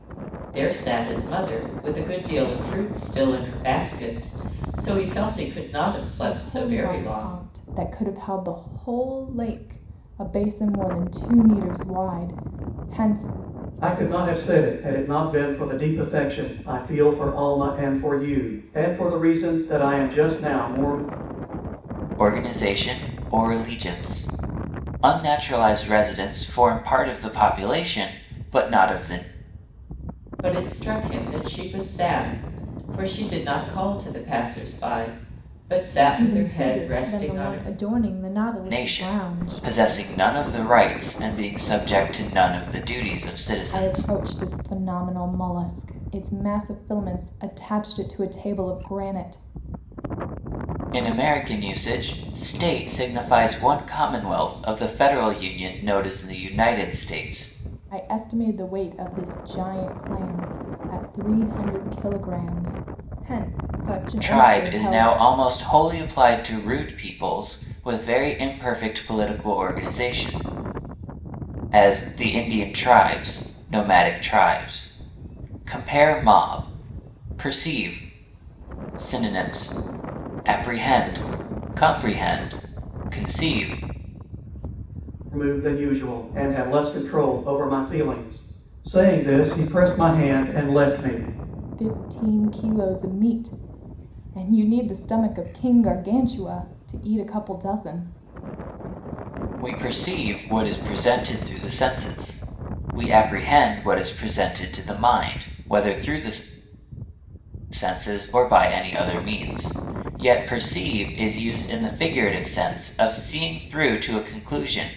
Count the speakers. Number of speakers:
4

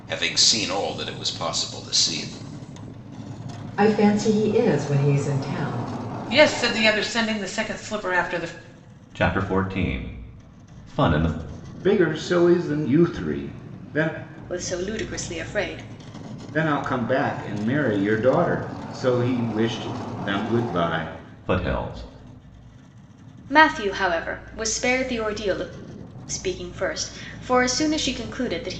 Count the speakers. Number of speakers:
6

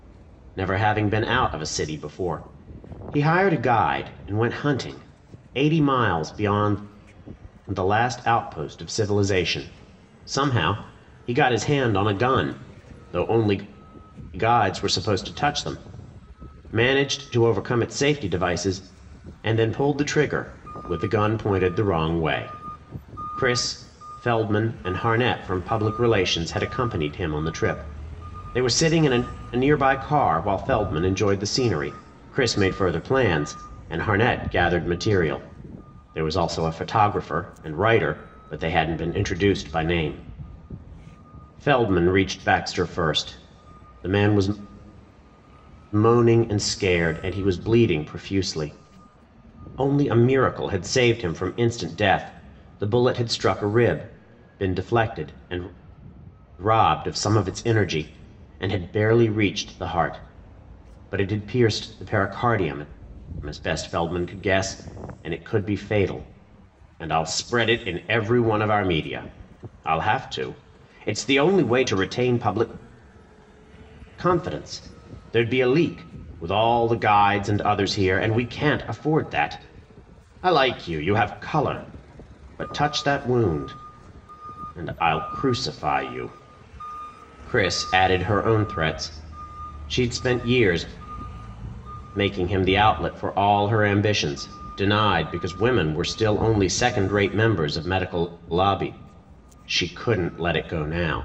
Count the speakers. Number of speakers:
1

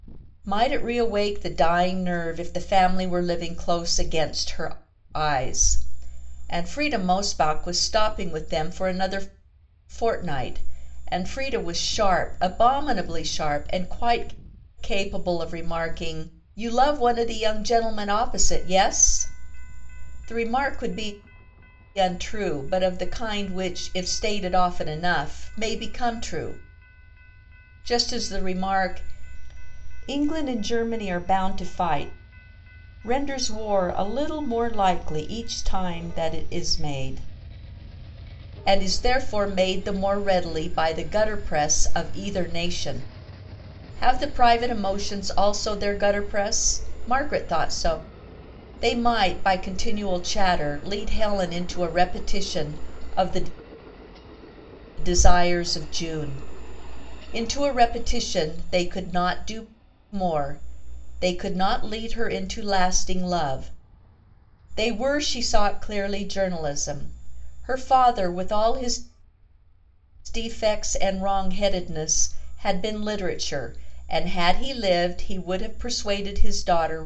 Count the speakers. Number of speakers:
1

